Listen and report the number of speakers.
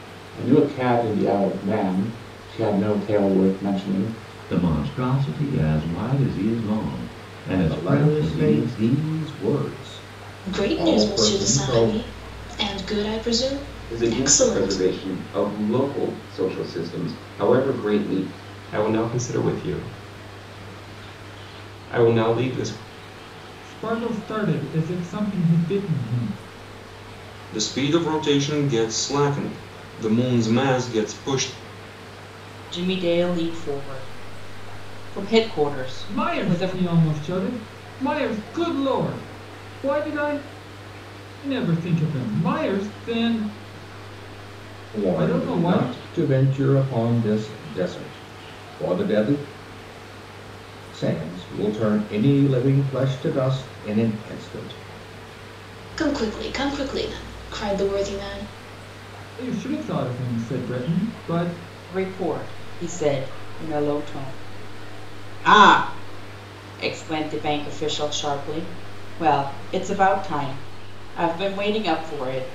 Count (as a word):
nine